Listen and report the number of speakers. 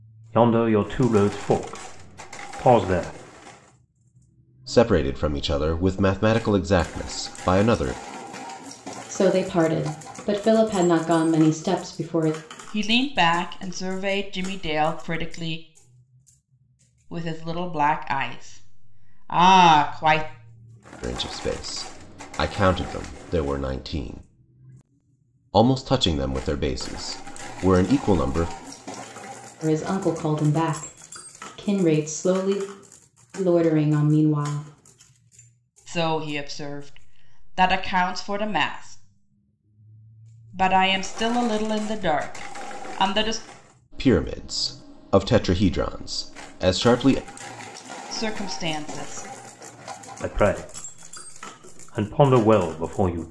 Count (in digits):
4